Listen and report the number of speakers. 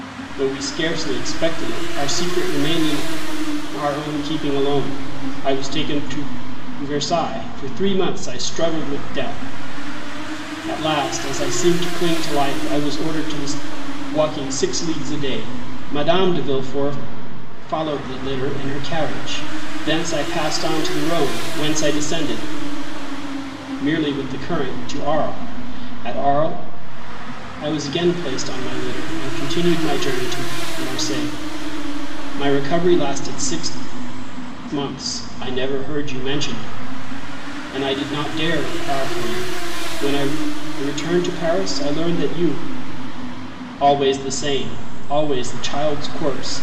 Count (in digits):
1